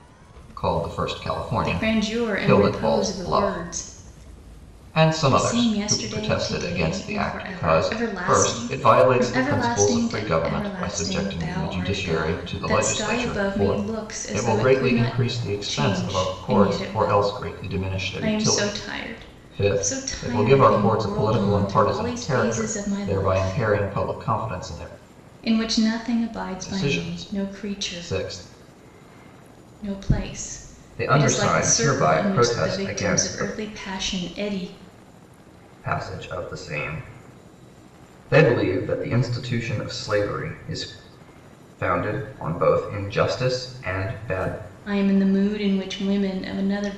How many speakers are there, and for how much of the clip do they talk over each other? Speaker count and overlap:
2, about 48%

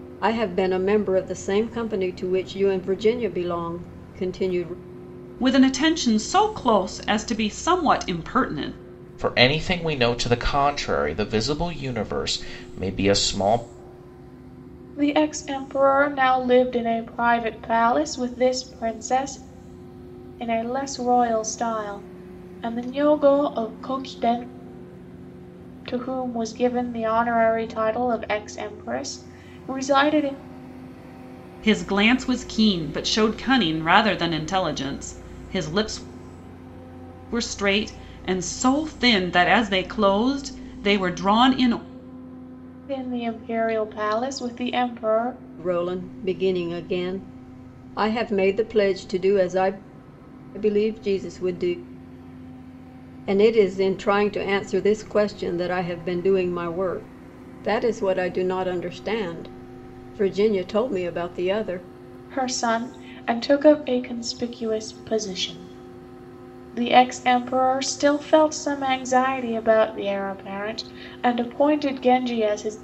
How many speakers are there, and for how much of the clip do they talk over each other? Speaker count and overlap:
4, no overlap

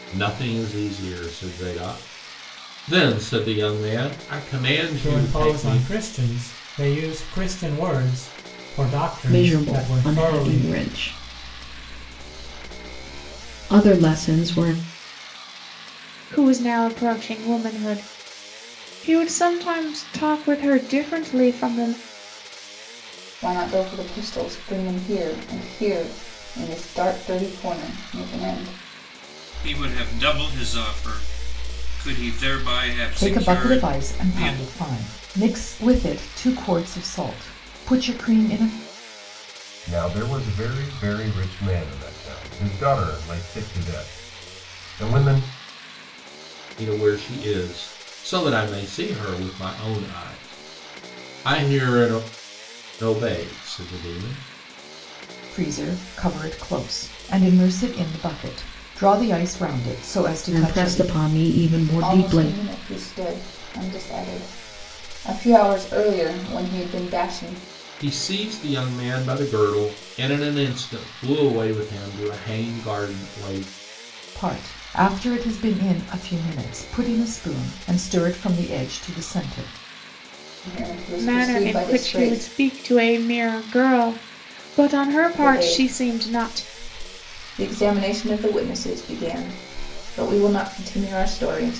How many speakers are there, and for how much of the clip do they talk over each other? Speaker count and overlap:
8, about 8%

